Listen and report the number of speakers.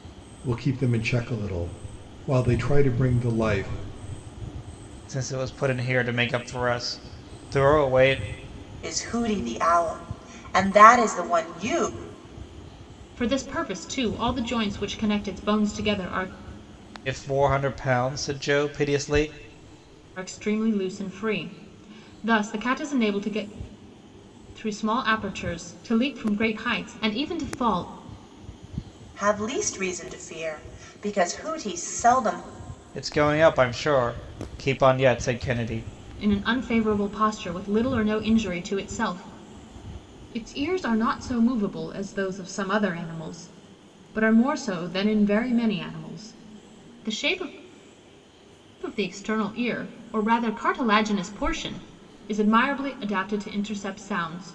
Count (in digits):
4